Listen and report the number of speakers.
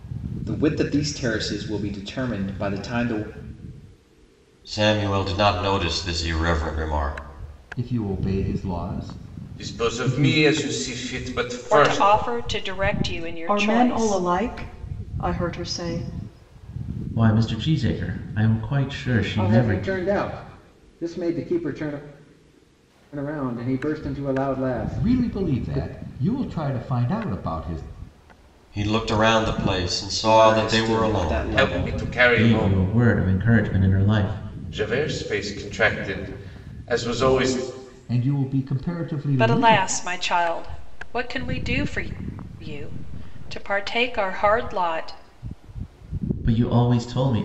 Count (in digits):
8